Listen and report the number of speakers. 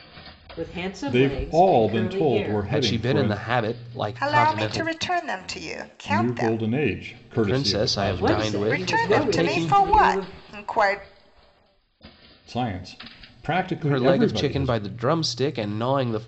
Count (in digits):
4